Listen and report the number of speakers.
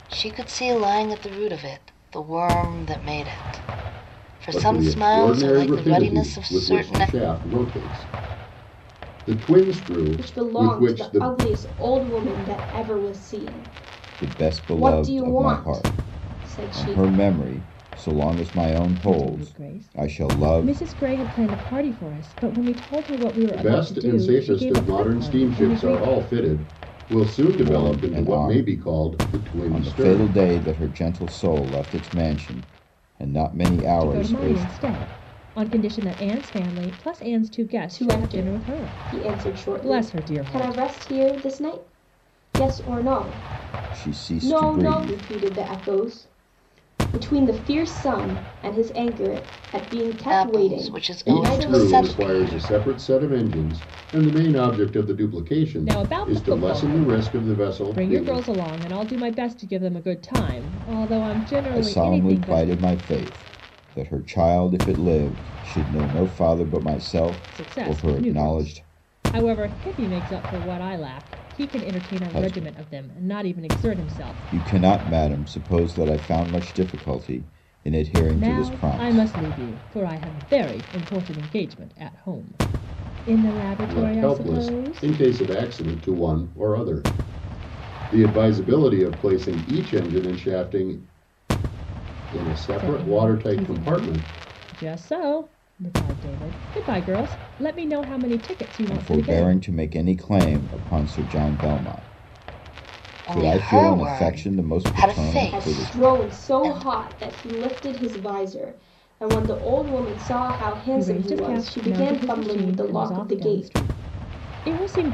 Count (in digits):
5